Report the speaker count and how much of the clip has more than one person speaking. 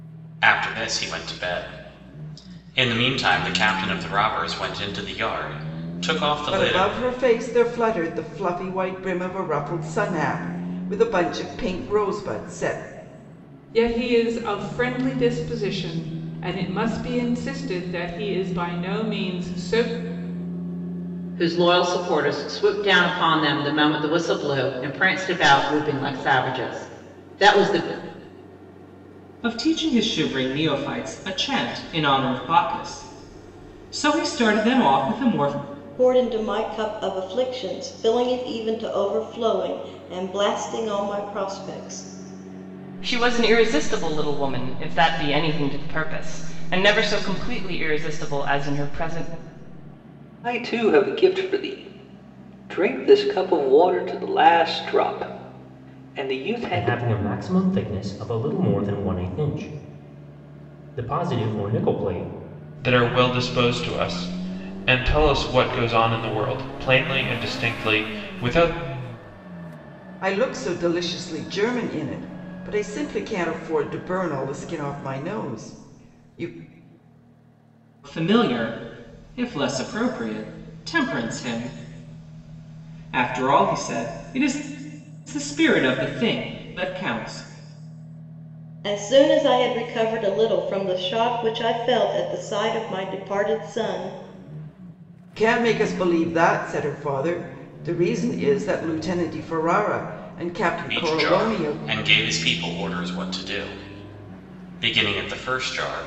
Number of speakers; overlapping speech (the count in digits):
10, about 2%